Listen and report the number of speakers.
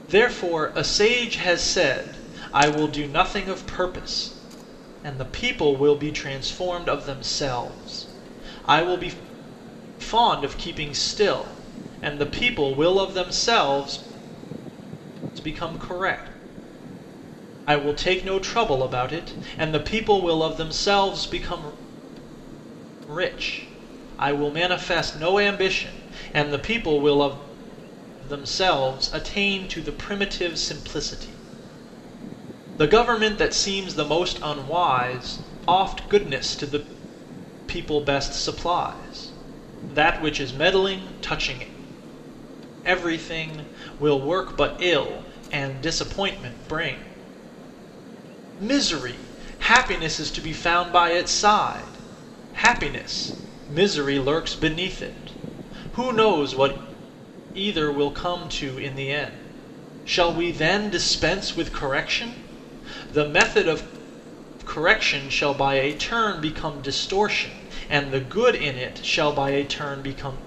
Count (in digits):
1